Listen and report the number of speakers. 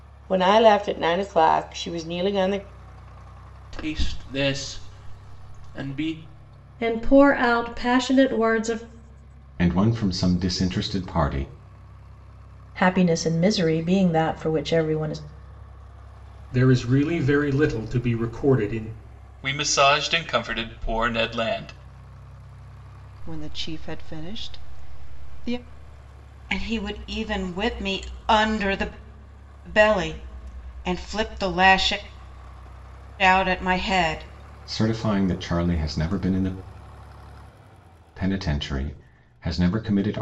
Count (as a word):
nine